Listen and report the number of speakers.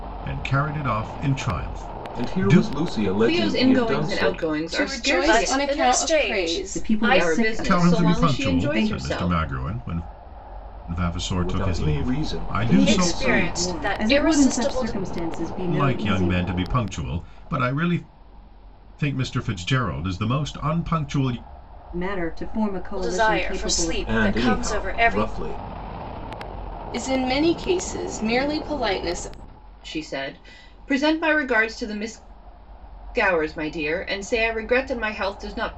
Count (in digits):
6